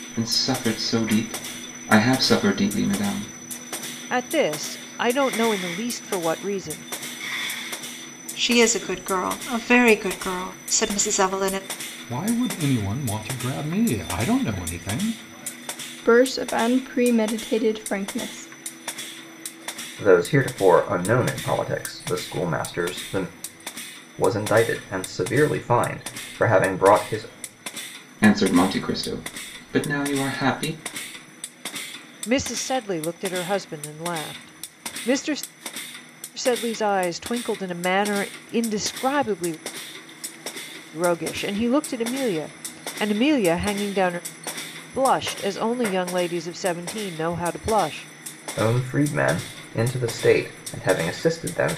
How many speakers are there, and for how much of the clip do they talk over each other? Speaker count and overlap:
6, no overlap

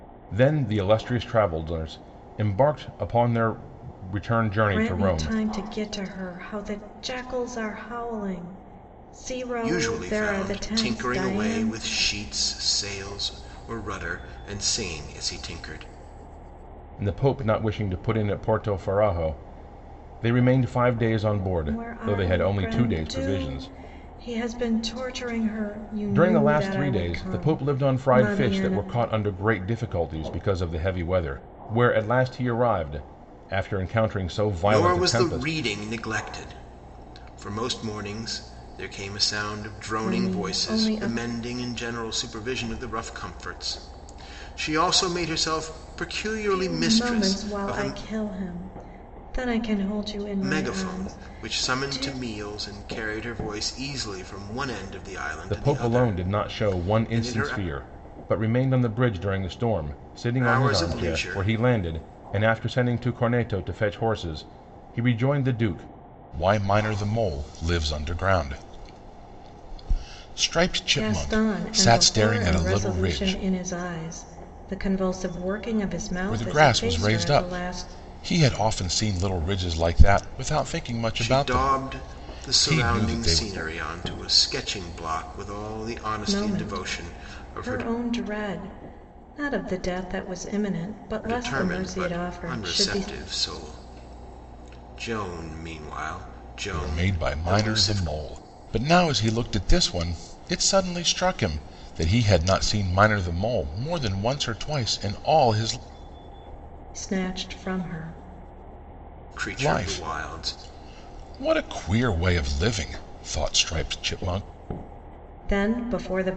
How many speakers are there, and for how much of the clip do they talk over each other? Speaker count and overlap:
3, about 25%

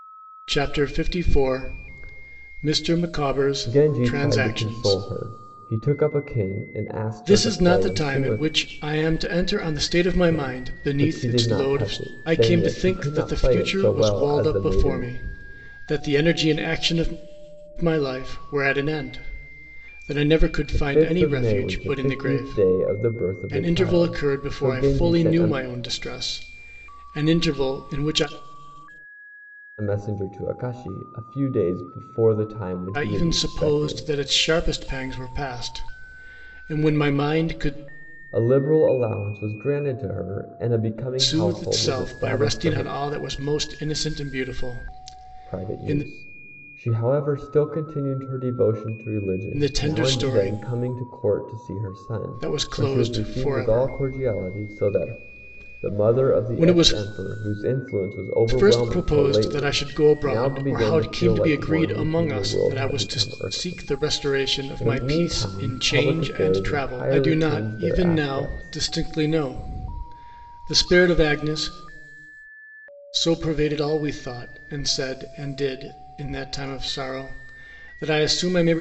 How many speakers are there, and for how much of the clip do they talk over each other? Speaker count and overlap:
2, about 38%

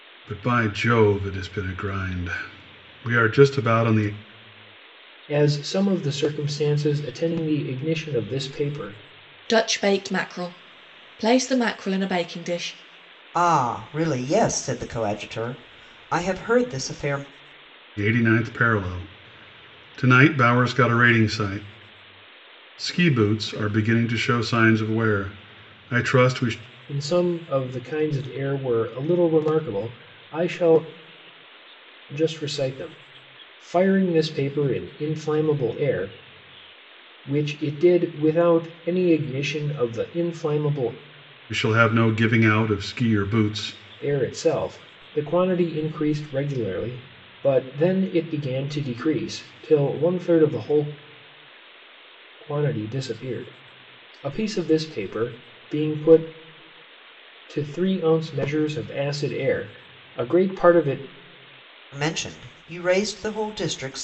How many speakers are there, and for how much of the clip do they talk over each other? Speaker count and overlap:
4, no overlap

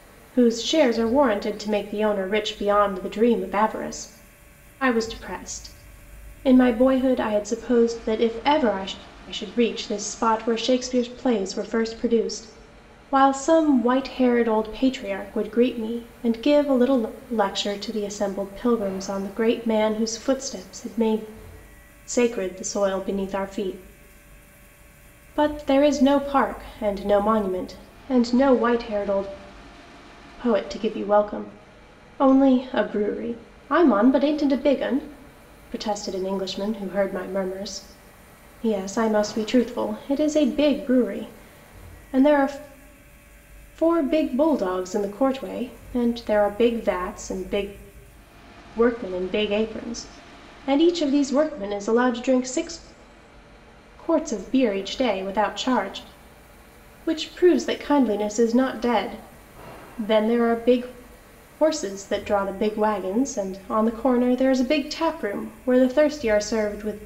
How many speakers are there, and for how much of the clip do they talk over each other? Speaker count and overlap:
1, no overlap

